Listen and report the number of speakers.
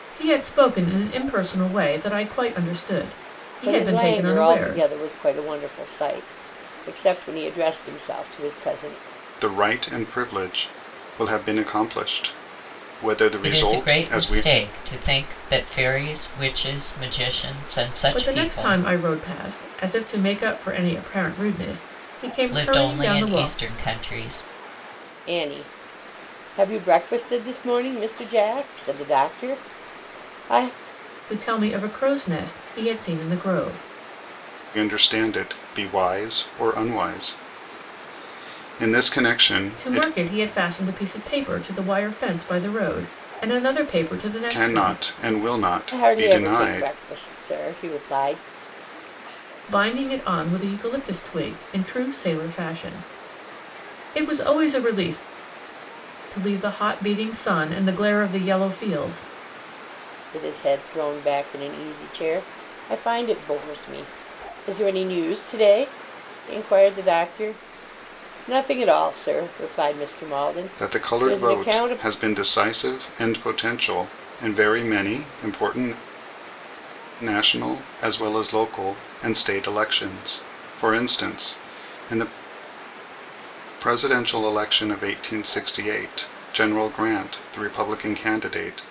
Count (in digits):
4